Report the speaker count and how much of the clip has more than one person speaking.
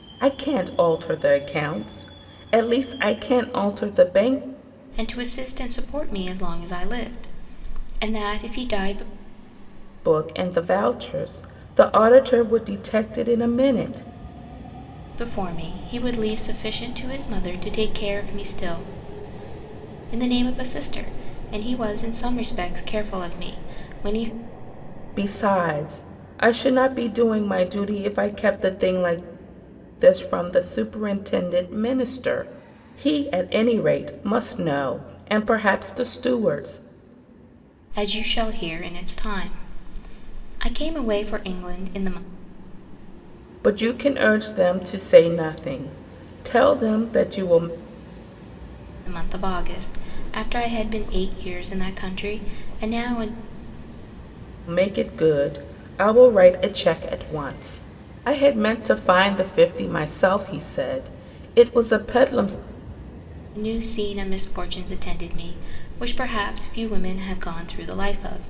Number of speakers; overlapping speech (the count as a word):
two, no overlap